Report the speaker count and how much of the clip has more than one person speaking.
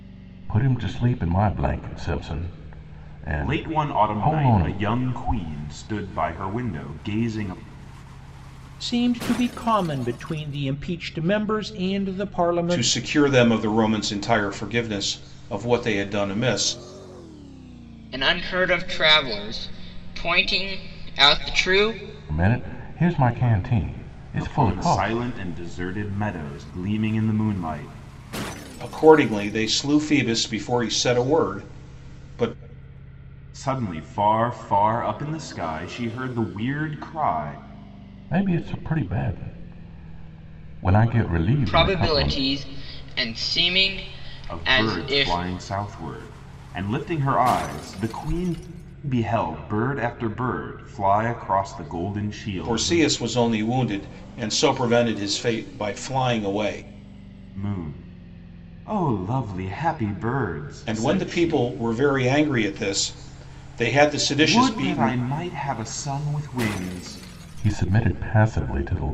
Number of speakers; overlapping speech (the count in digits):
5, about 9%